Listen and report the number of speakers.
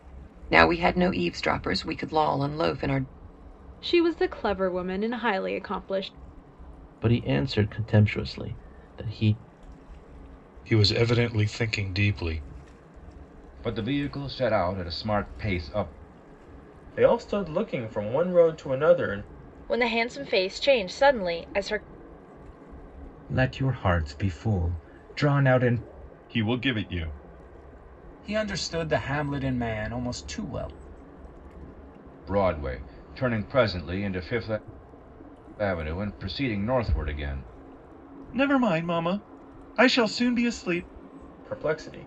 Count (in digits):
10